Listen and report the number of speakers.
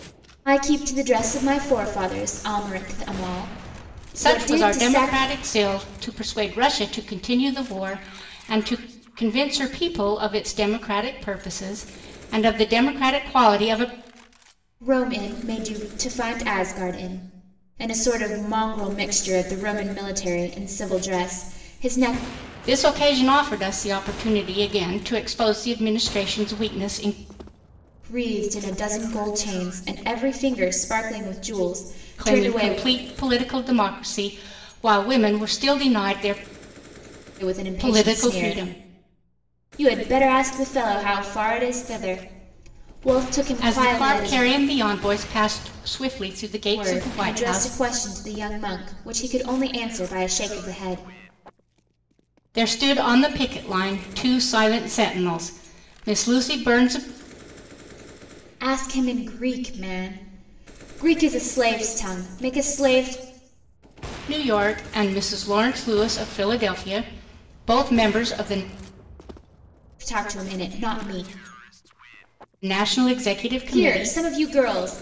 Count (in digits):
2